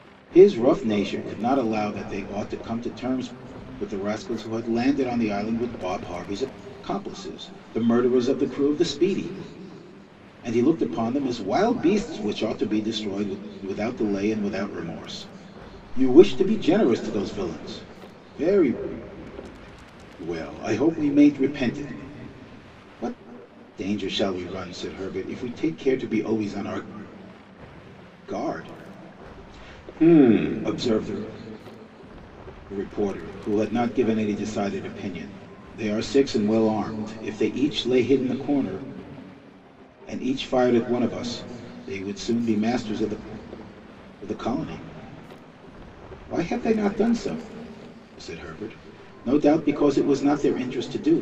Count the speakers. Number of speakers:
1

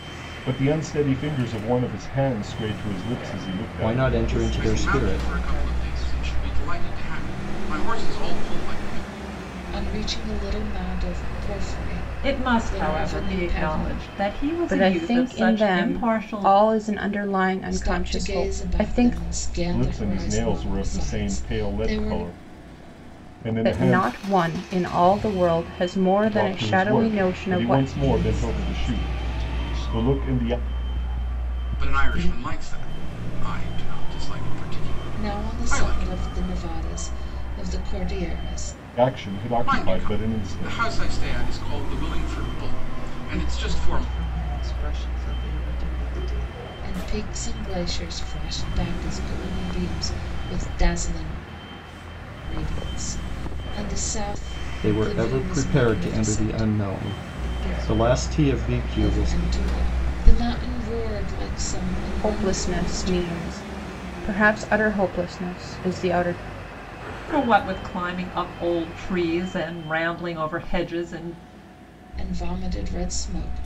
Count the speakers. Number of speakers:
7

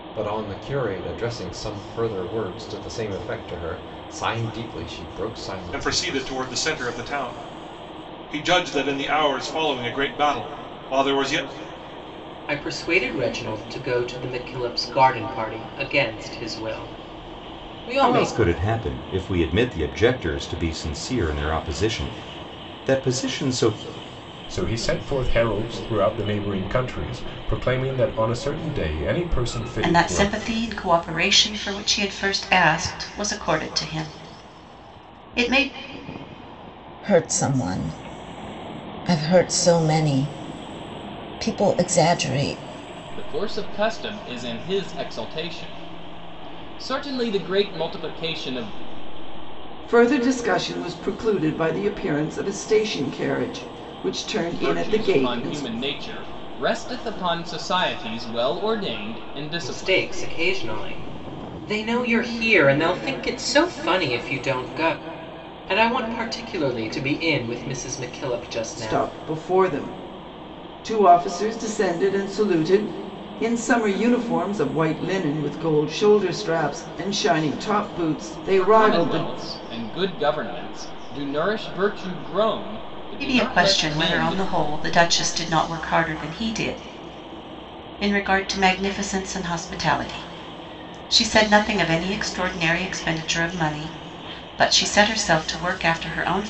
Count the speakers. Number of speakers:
9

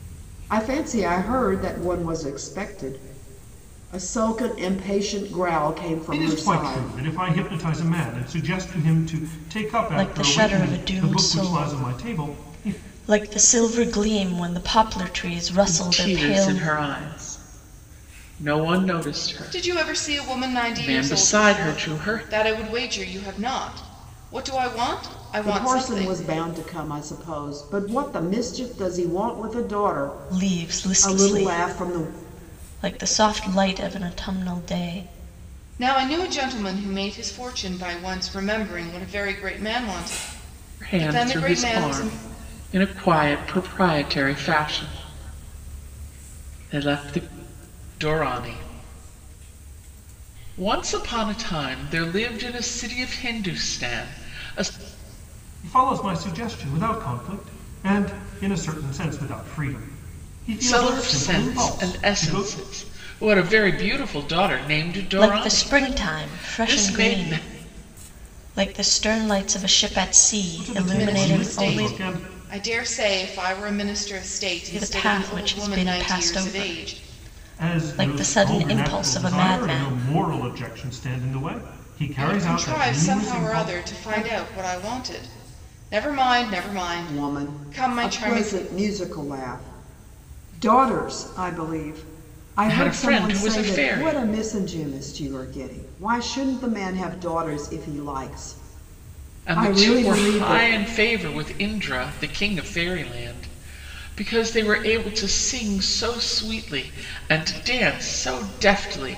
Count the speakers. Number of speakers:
5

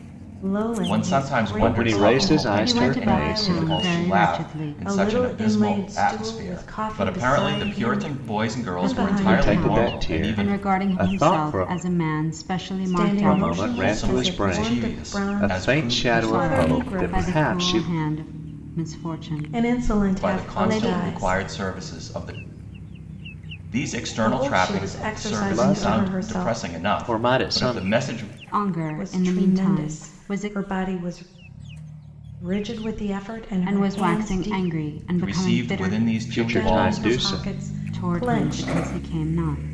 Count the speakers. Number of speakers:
4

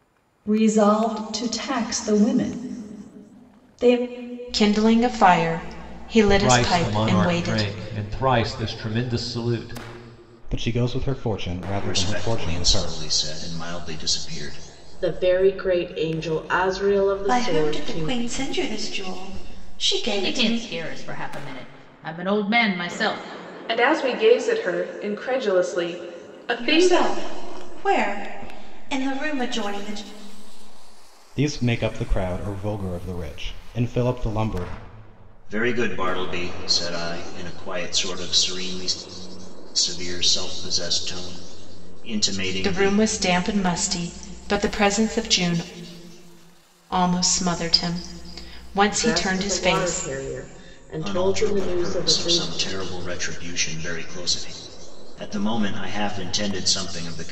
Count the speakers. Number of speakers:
9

